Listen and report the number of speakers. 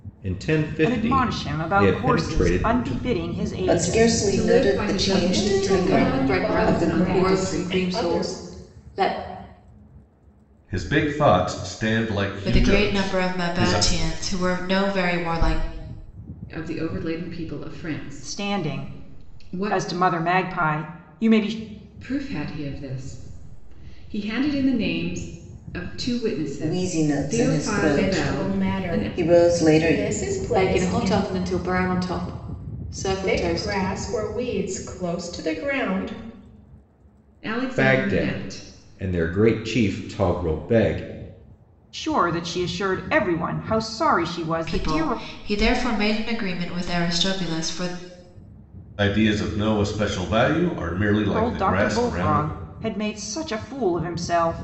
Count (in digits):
8